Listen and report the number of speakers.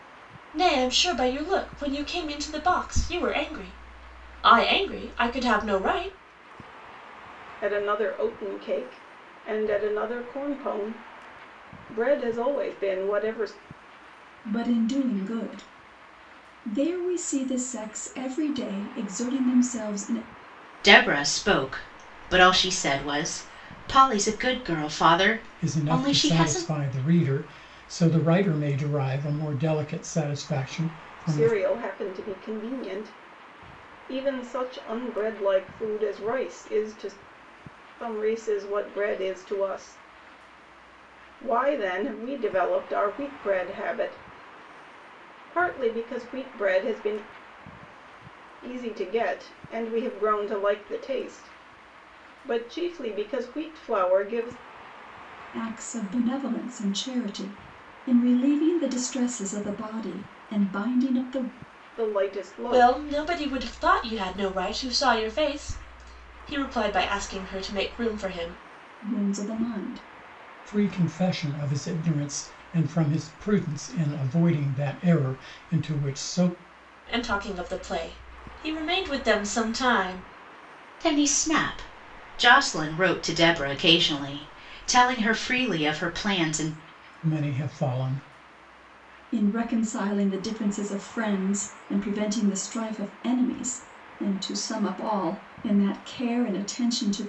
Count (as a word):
five